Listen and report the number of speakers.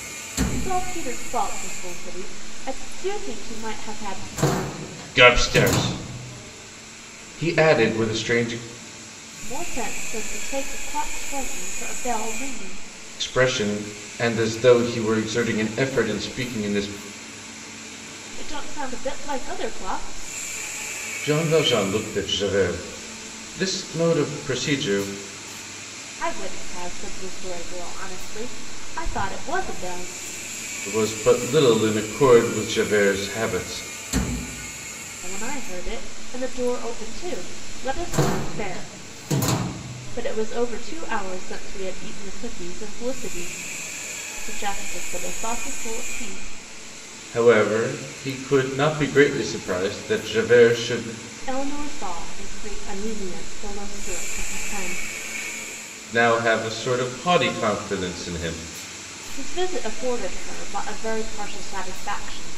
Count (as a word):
two